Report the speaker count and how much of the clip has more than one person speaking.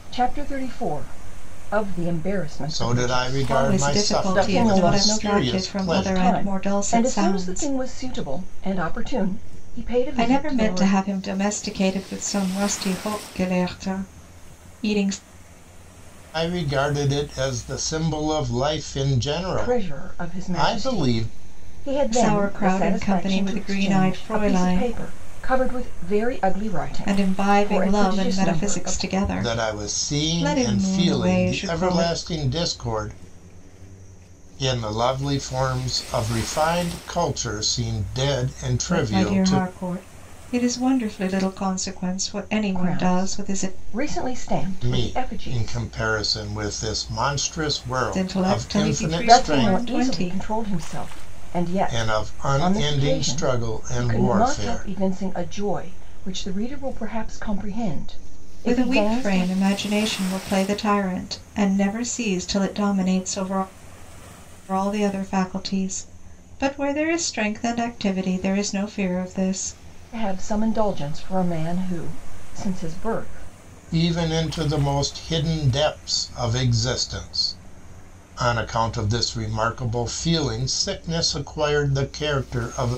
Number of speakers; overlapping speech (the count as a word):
three, about 29%